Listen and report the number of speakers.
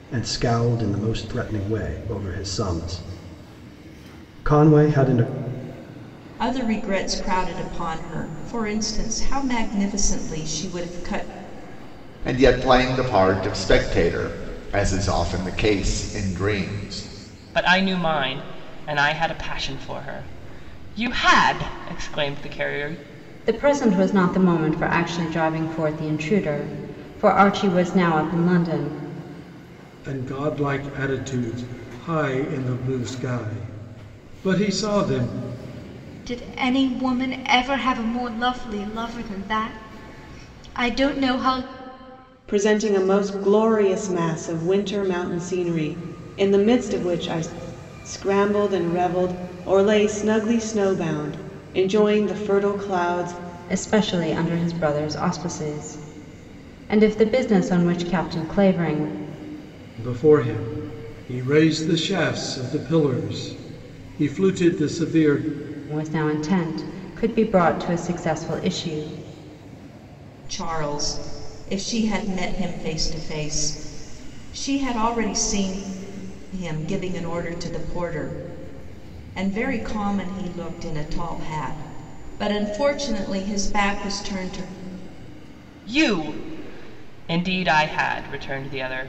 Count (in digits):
8